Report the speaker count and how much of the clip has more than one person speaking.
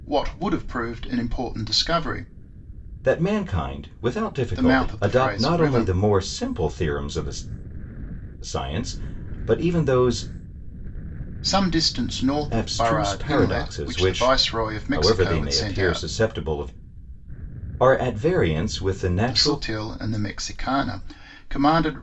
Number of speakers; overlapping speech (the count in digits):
2, about 23%